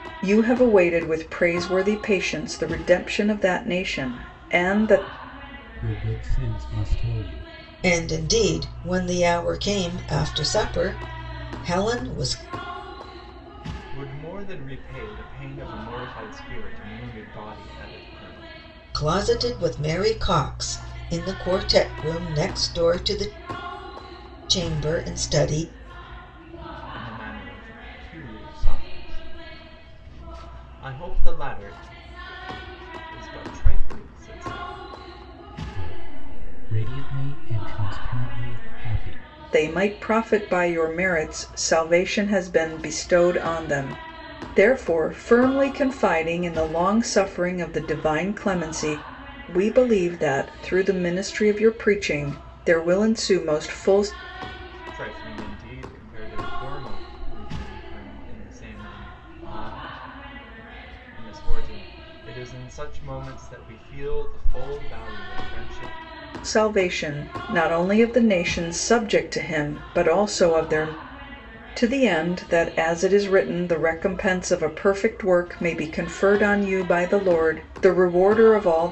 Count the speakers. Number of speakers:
4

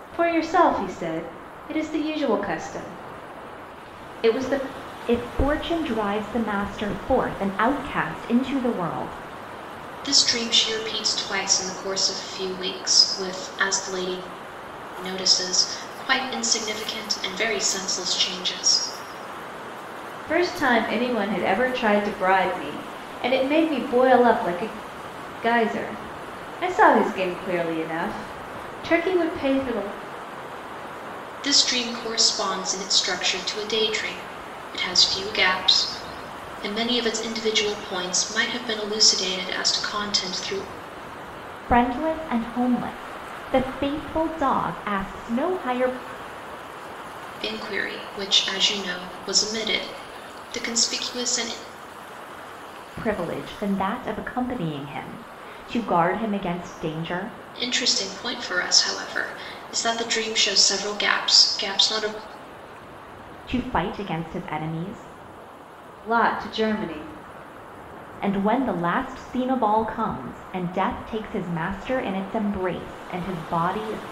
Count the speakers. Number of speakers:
3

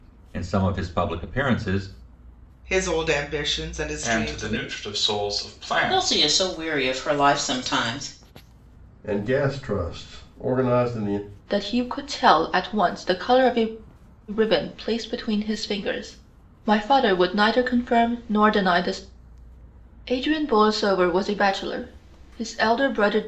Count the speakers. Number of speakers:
6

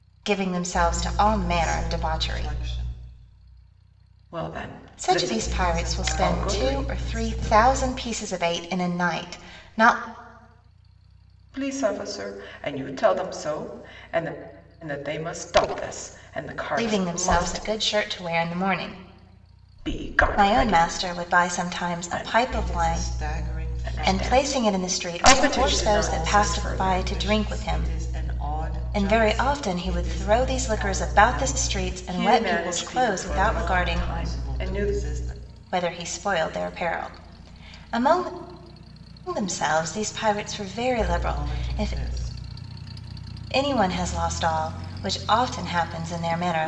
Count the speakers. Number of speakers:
3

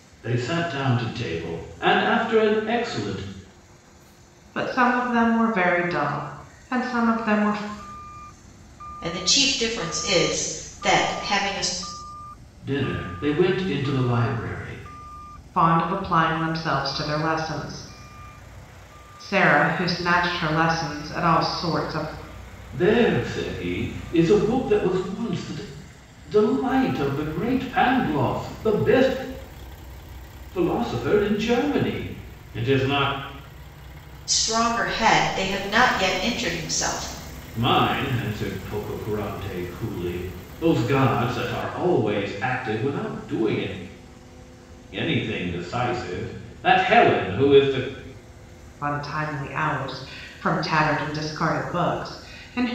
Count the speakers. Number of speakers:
3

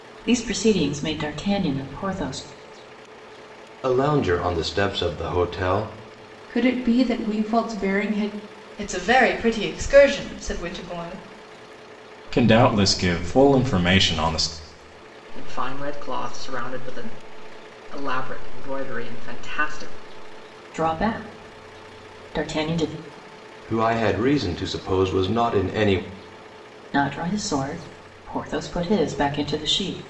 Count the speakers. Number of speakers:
6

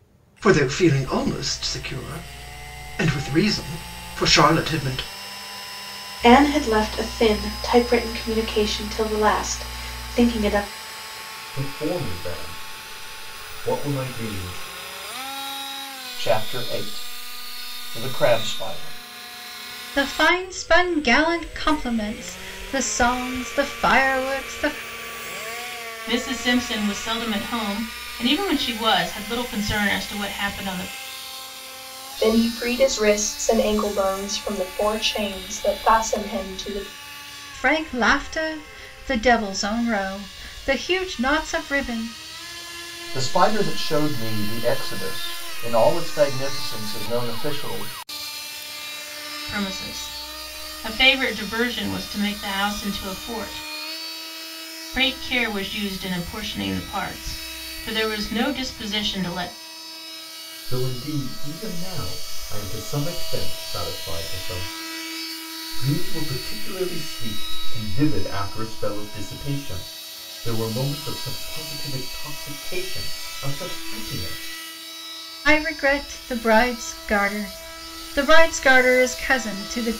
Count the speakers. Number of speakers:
7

